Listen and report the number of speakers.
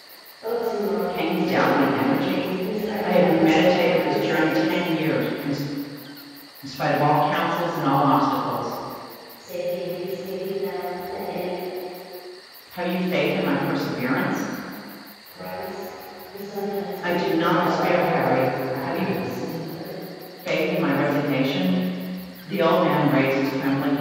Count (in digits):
2